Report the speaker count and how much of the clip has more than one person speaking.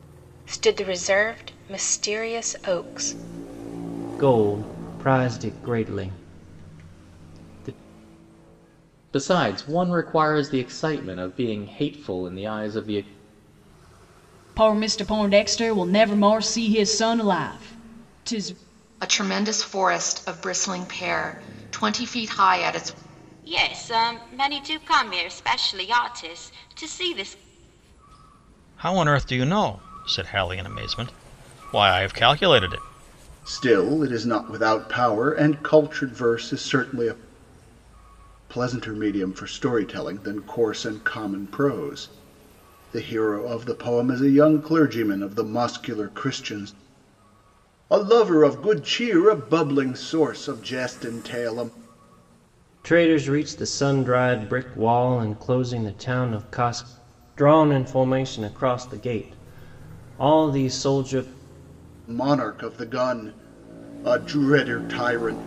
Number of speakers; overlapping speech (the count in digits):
8, no overlap